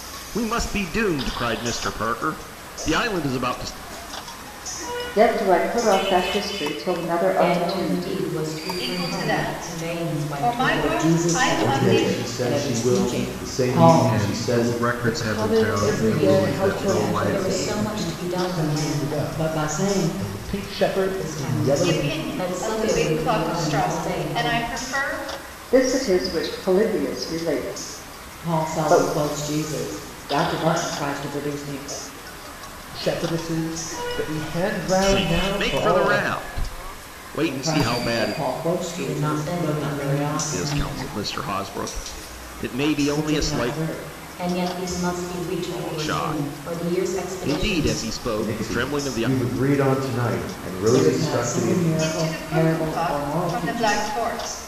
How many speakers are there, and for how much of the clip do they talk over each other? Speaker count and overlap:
8, about 50%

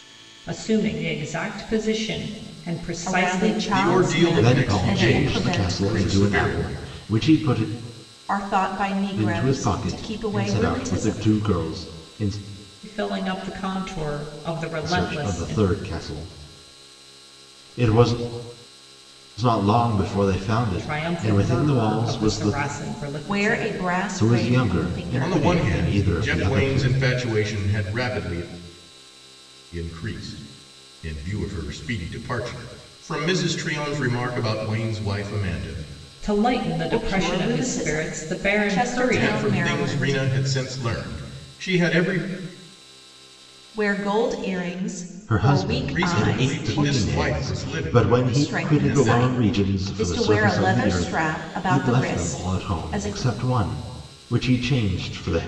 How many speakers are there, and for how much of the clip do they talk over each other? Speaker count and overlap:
4, about 41%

